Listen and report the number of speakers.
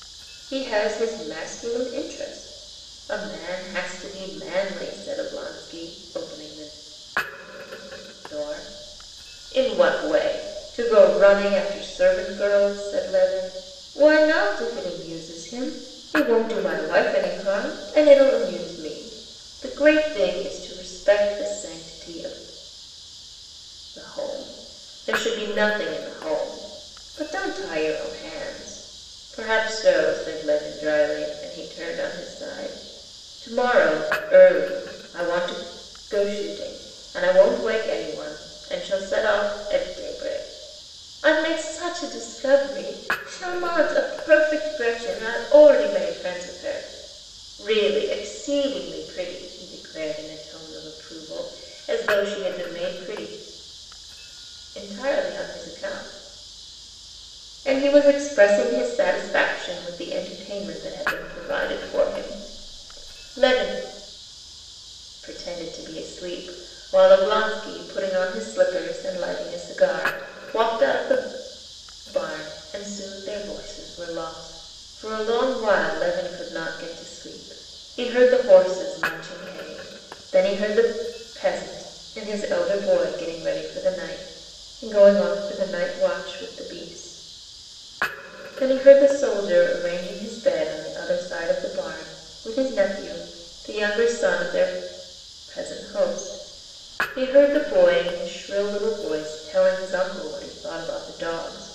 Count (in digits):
1